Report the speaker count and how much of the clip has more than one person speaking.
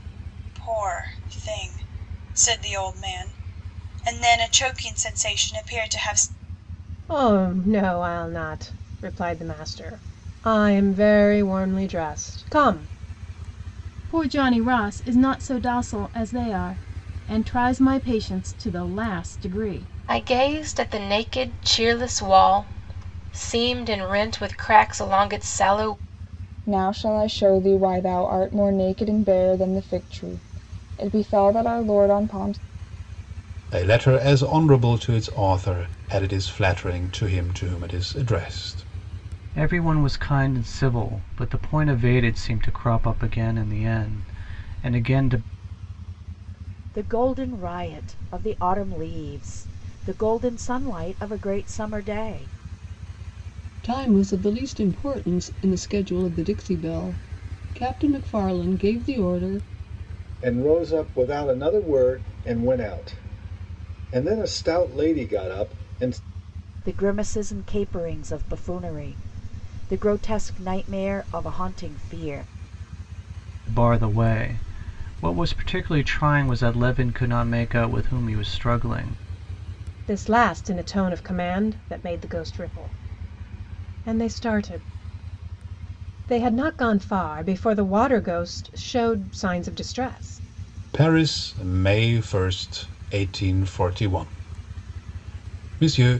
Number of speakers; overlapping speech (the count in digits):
10, no overlap